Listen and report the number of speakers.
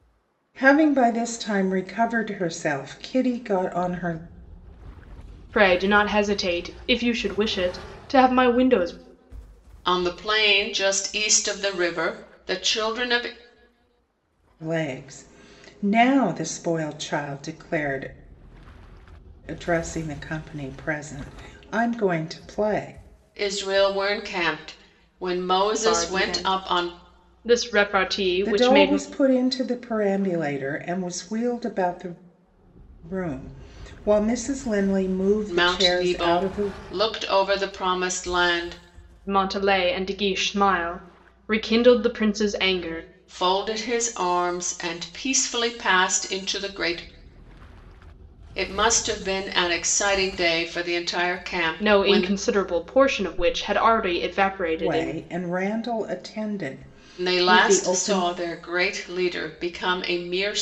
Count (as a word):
three